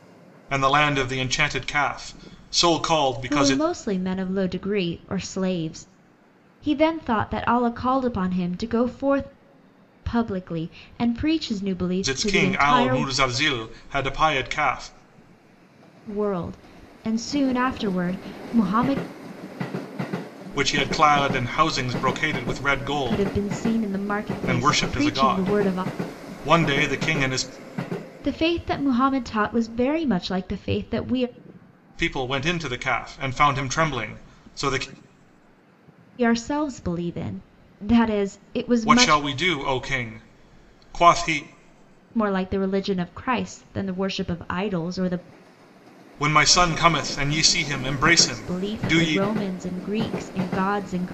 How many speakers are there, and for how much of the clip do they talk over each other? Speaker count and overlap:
two, about 9%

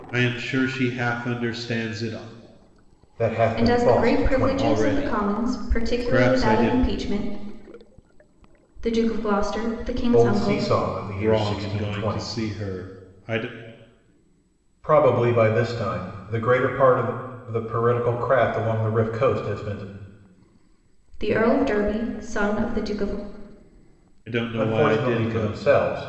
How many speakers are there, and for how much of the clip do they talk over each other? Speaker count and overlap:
three, about 23%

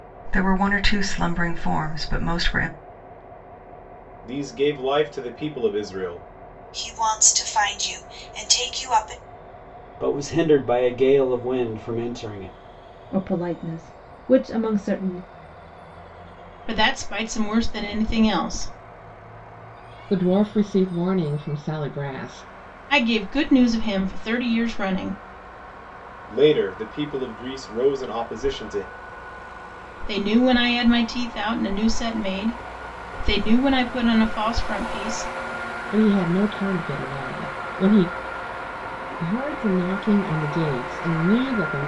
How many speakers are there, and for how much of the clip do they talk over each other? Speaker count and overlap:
seven, no overlap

